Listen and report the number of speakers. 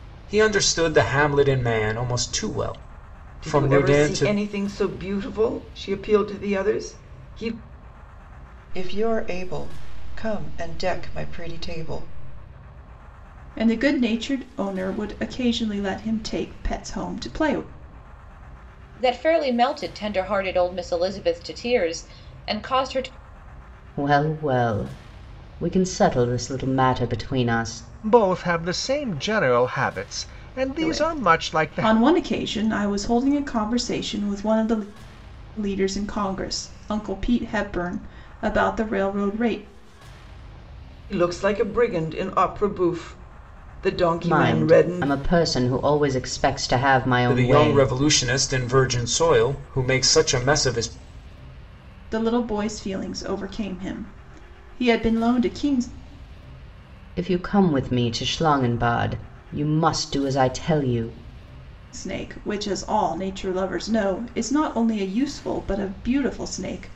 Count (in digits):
7